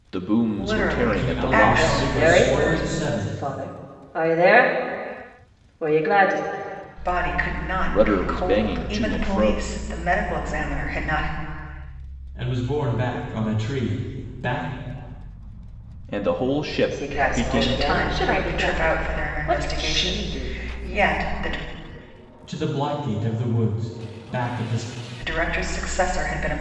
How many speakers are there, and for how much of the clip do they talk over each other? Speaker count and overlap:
four, about 30%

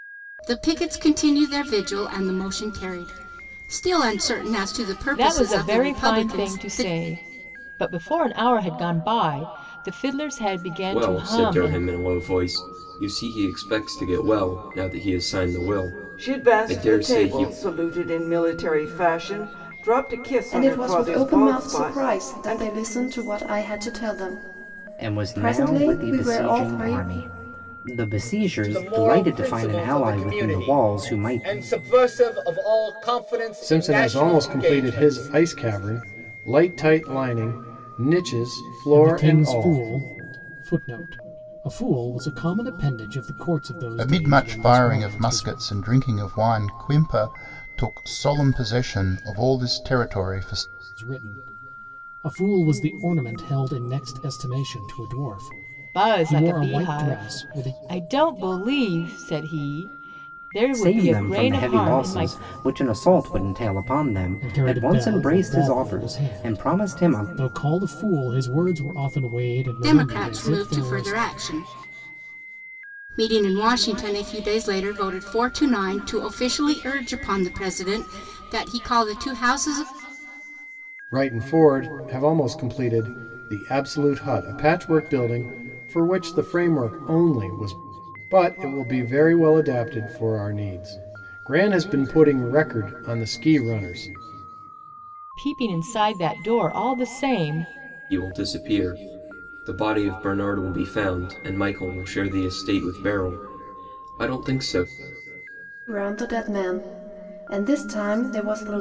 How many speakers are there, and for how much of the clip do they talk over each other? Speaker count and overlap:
ten, about 22%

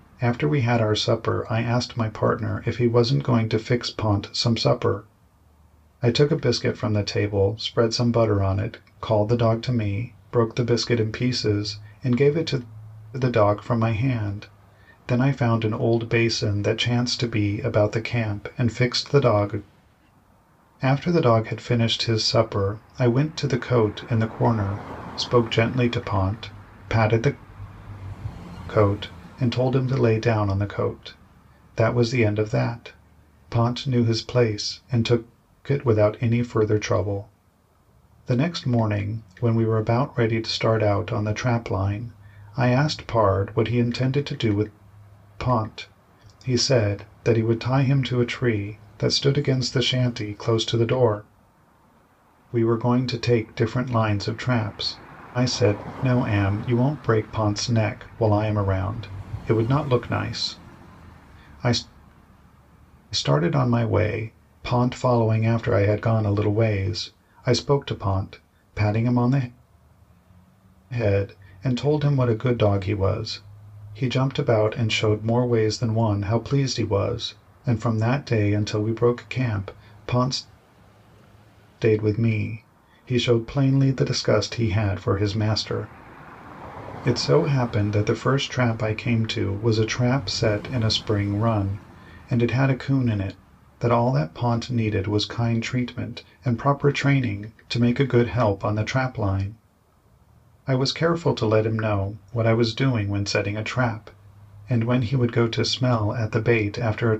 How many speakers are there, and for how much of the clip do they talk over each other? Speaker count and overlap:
one, no overlap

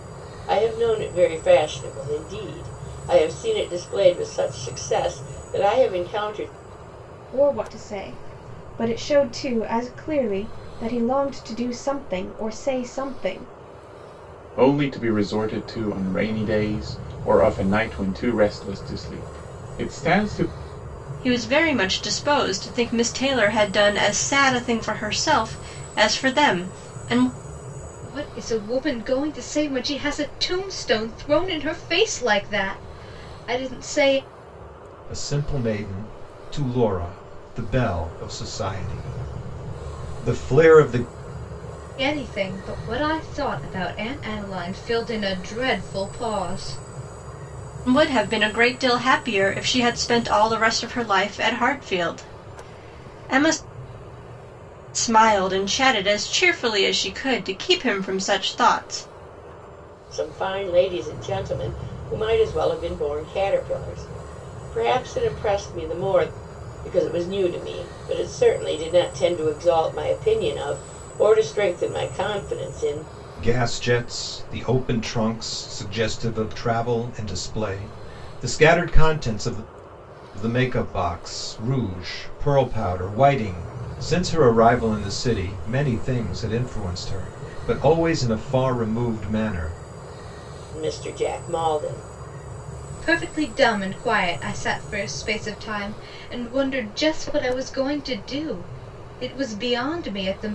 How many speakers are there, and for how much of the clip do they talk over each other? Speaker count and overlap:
six, no overlap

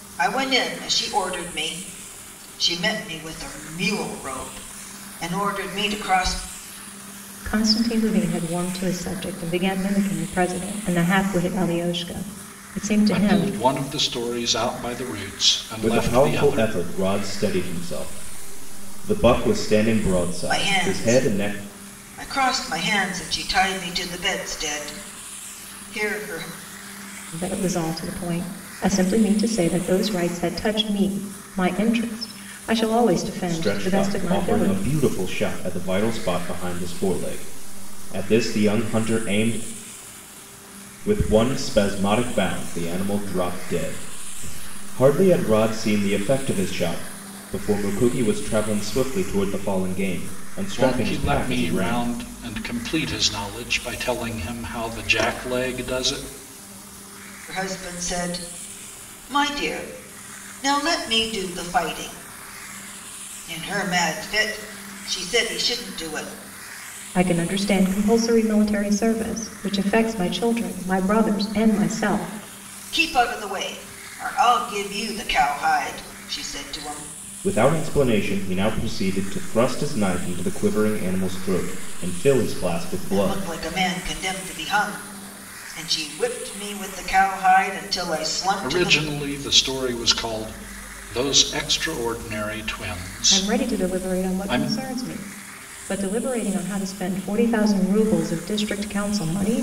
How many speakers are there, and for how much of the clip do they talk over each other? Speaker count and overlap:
four, about 8%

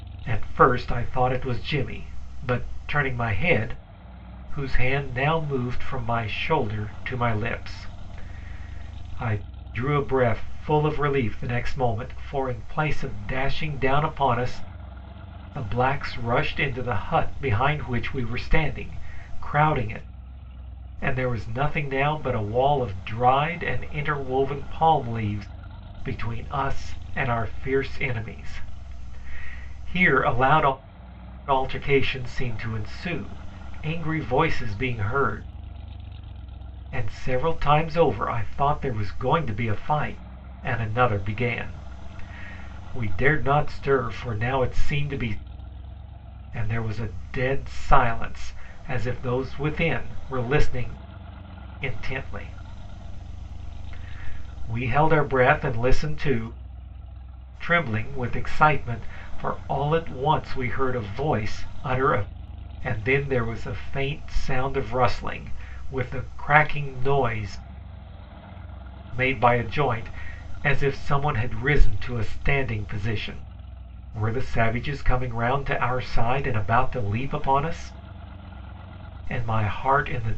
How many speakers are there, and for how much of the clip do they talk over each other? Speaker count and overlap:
one, no overlap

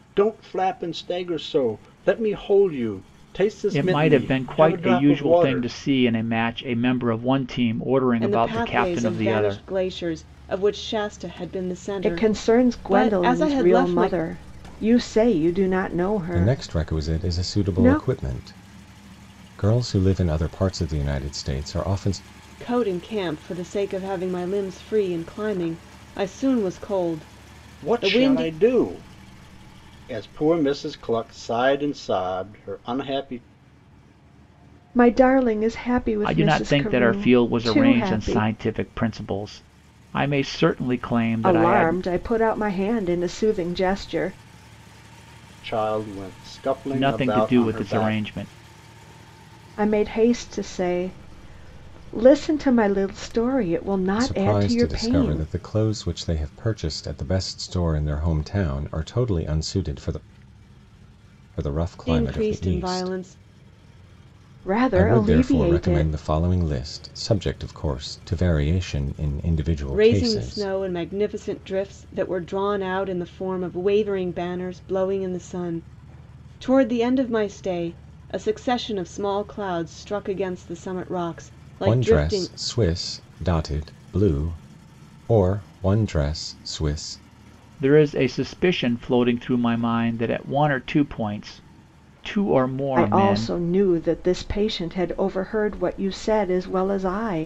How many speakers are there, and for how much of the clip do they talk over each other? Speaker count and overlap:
five, about 18%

